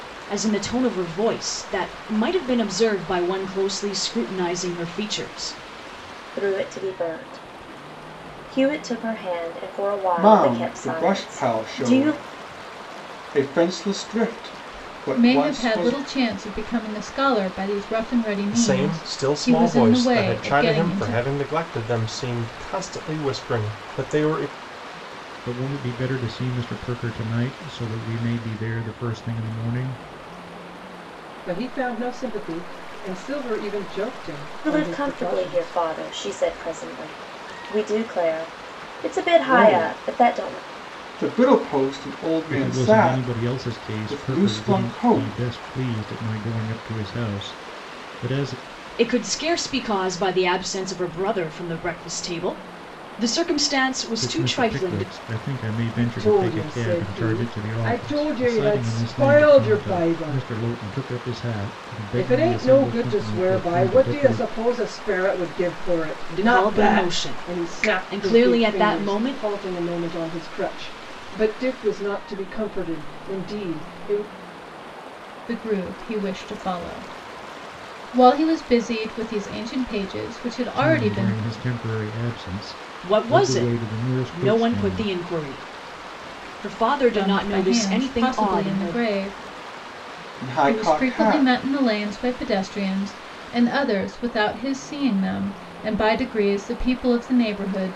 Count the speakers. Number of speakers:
7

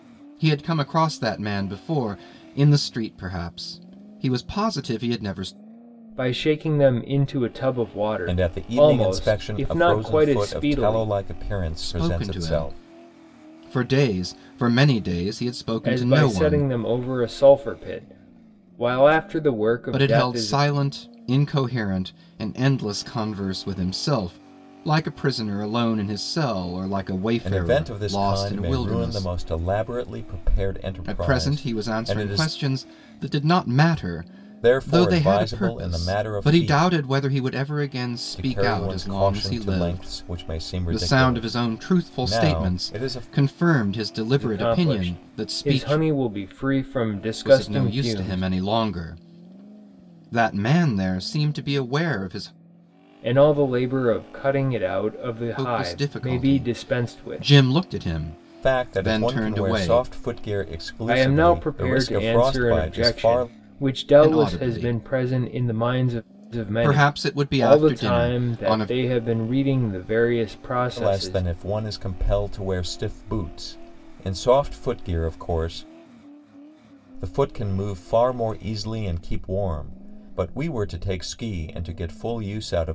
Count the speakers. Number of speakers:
3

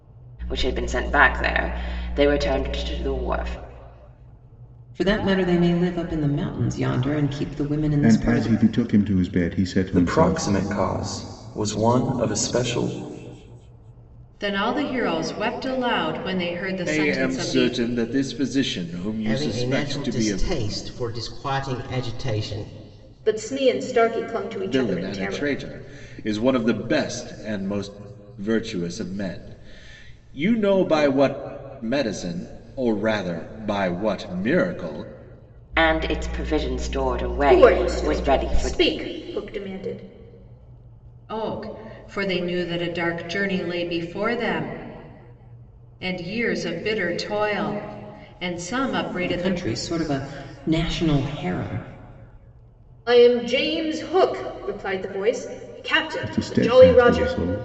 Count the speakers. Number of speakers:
8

